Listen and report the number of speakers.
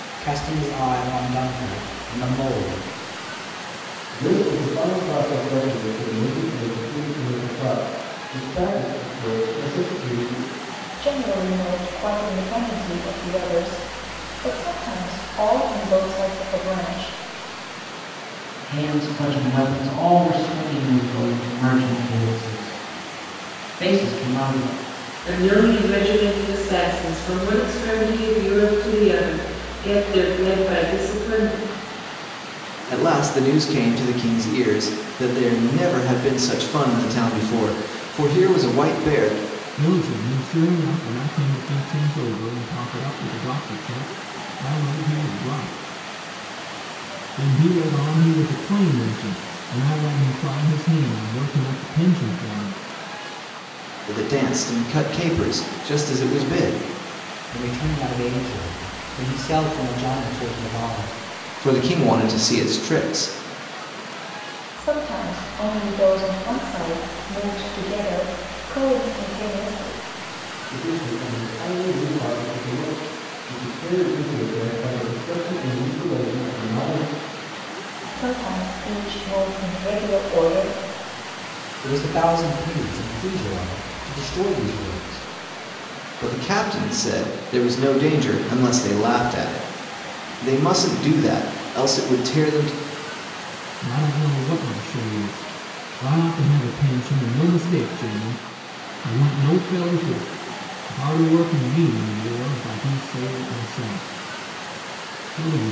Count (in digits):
7